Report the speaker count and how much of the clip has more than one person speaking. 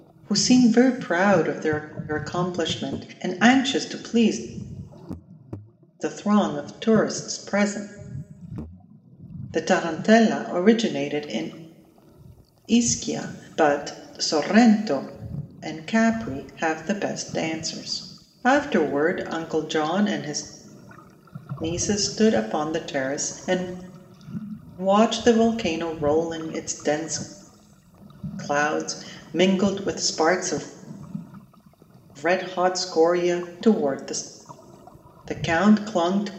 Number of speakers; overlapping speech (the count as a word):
one, no overlap